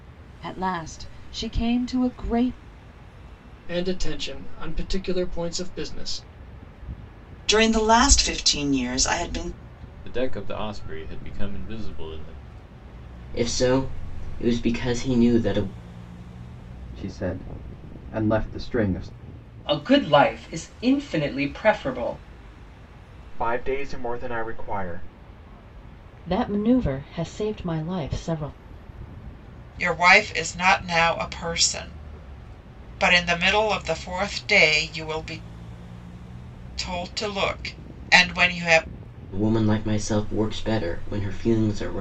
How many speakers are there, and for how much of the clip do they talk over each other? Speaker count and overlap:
10, no overlap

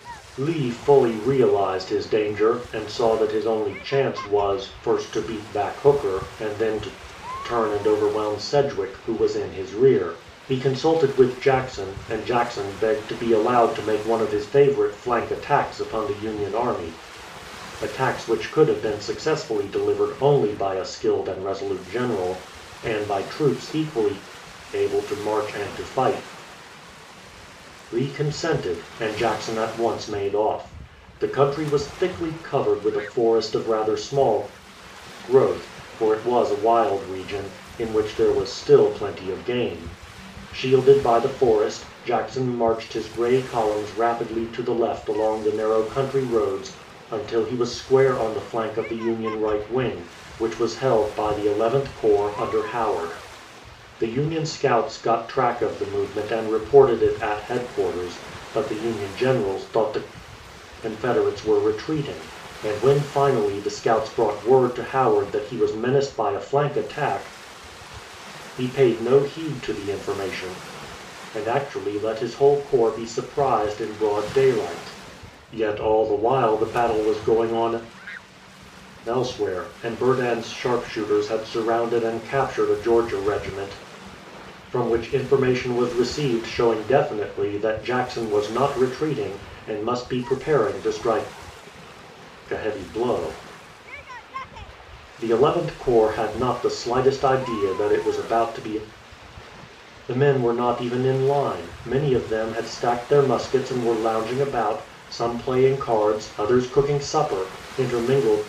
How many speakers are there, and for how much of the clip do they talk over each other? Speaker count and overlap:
1, no overlap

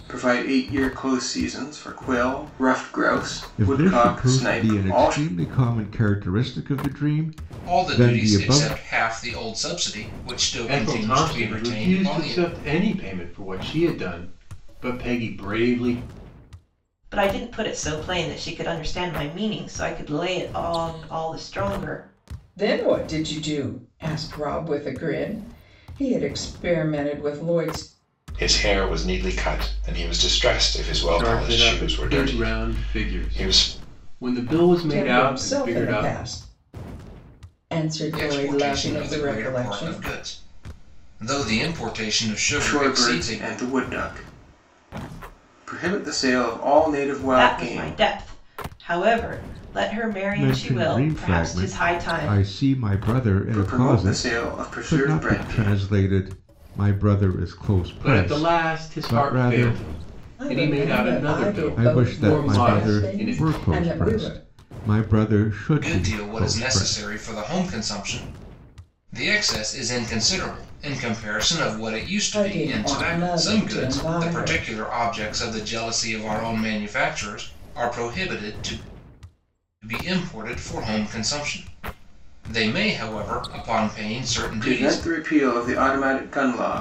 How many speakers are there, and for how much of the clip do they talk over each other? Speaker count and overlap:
7, about 30%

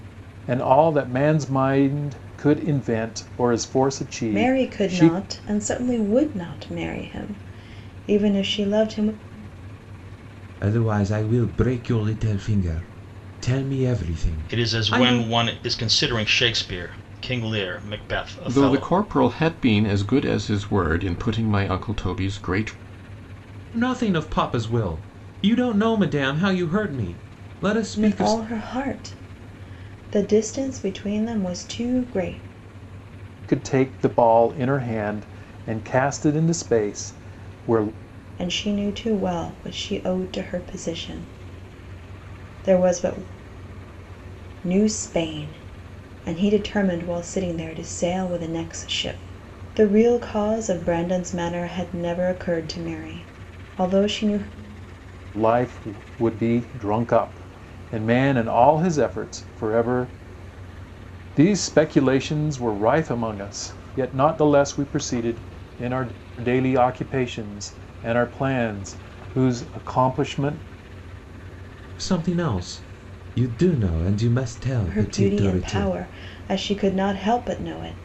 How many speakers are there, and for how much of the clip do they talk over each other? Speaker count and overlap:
5, about 5%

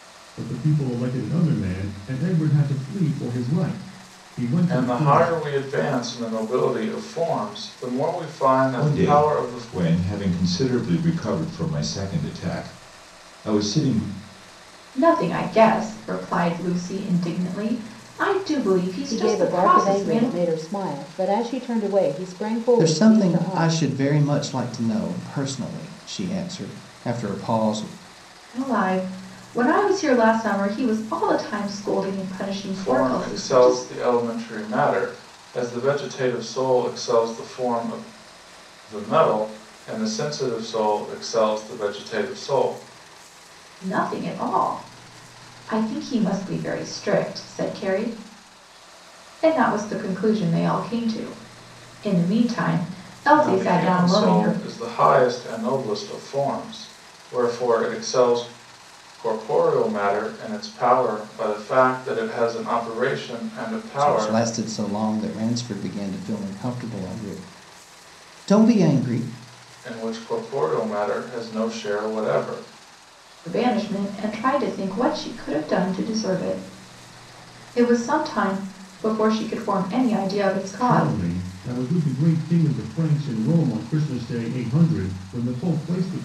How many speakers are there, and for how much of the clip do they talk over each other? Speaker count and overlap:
6, about 8%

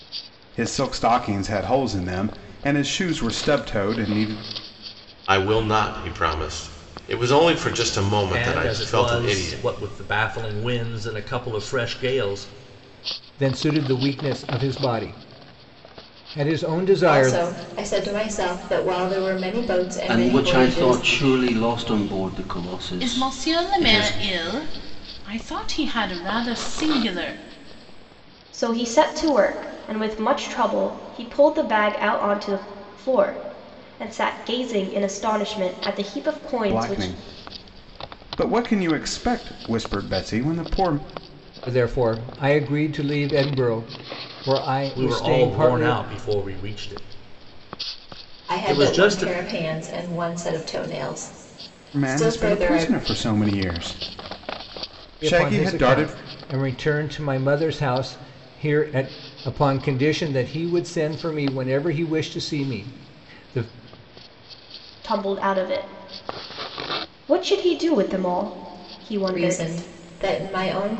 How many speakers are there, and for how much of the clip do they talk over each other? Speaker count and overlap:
8, about 12%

